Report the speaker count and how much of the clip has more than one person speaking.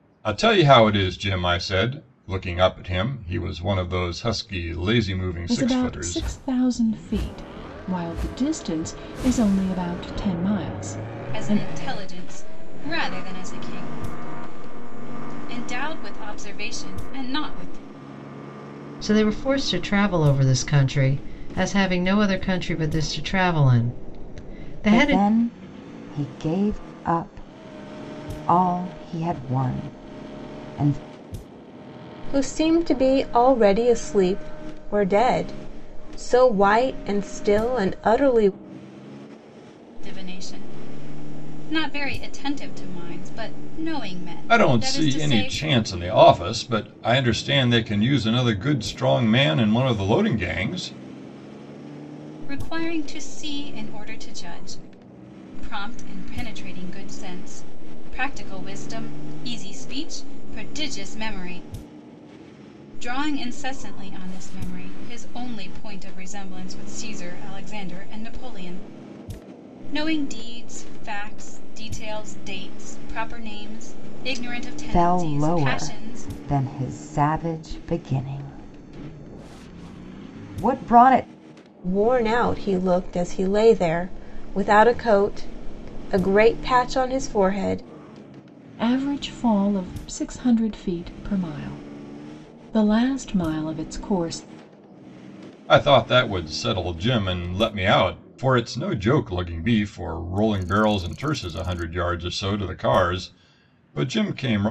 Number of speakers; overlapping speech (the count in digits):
6, about 4%